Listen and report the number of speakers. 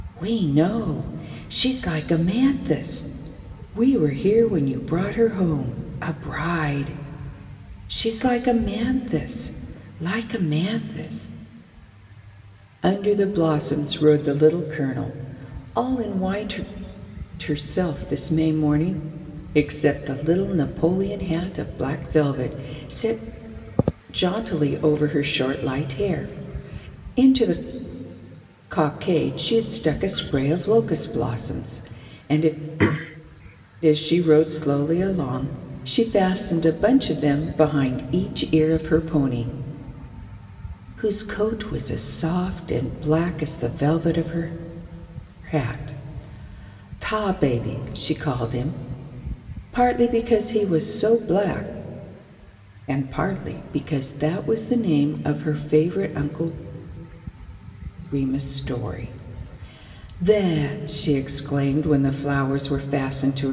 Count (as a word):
one